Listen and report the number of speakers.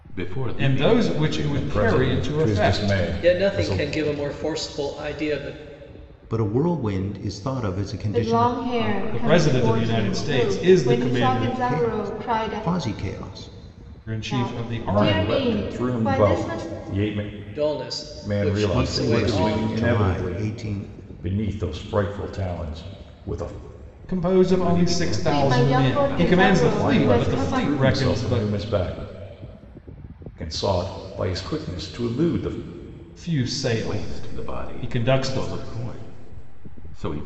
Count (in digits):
6